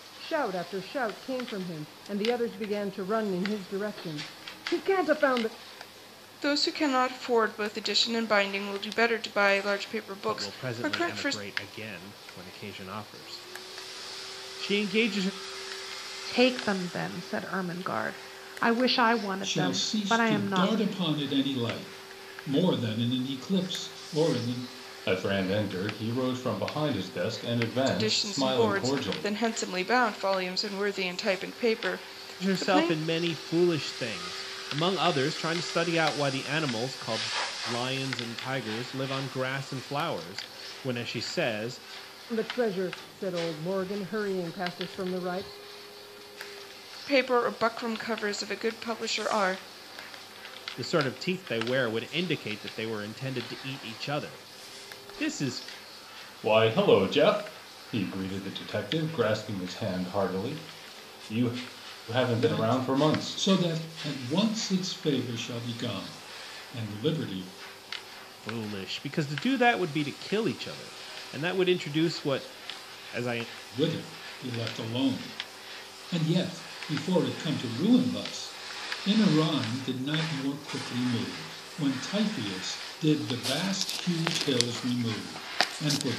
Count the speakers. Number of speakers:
6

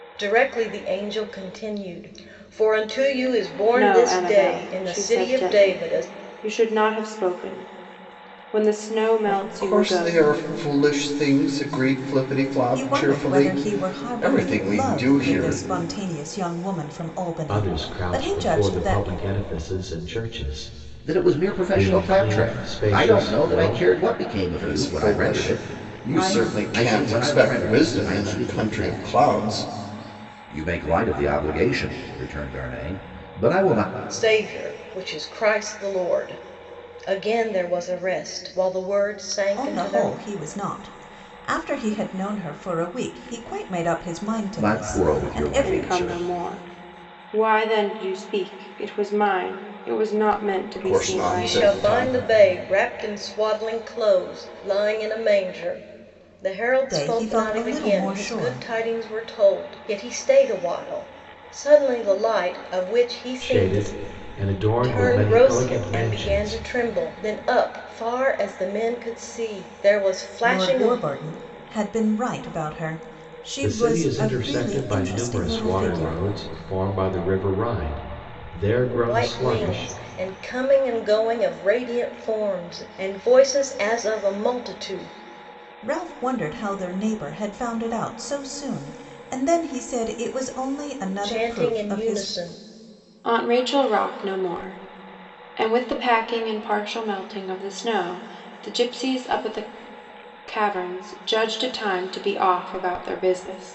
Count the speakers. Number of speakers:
6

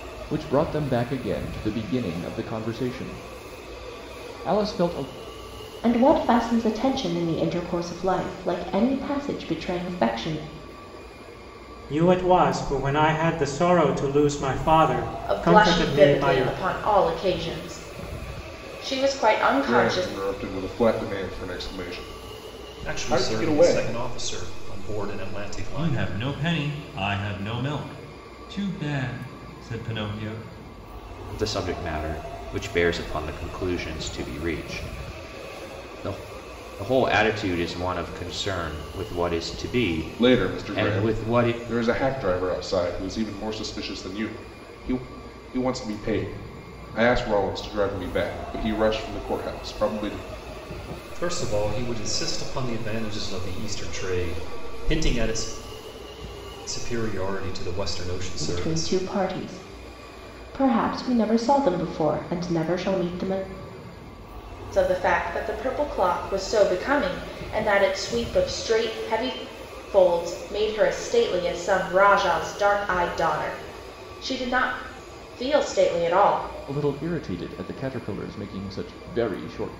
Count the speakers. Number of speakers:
8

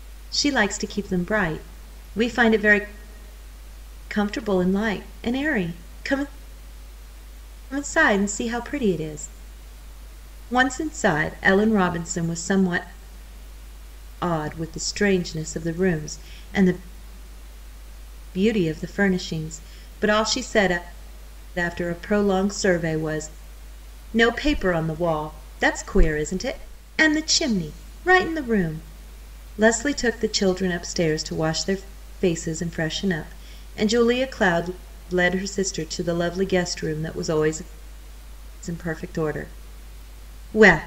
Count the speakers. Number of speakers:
1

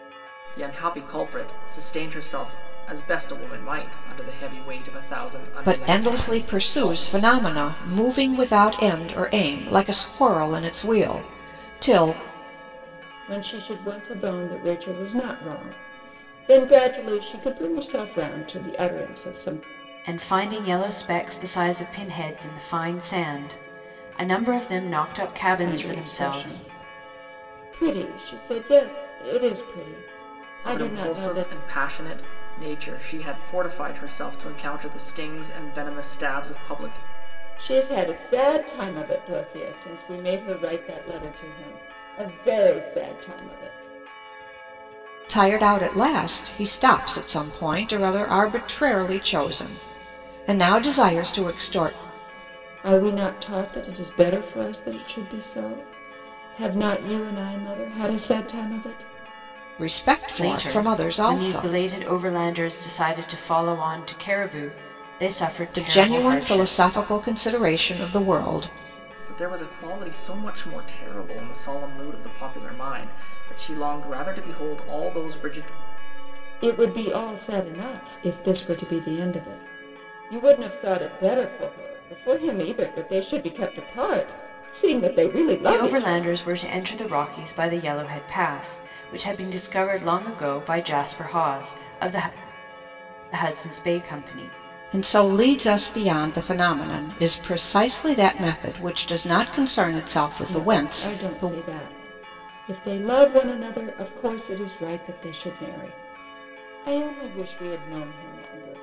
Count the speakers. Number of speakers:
4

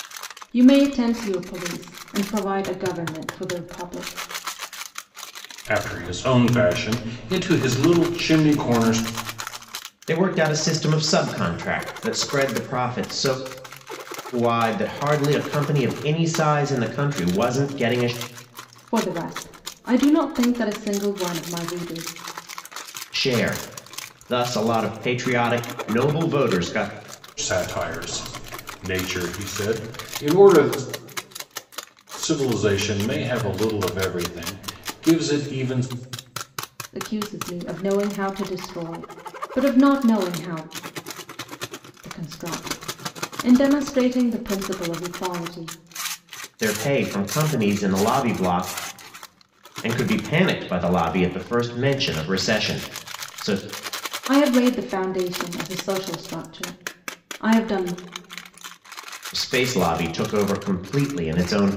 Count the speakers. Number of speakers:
3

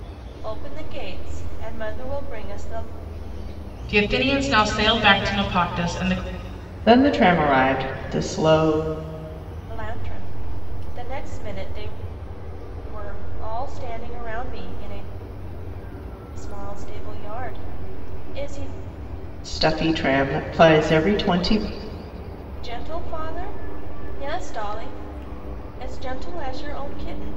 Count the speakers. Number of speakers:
3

